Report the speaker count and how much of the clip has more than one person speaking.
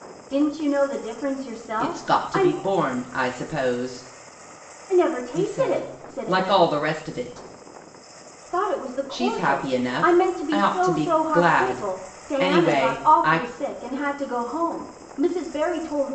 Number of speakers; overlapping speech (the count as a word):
two, about 40%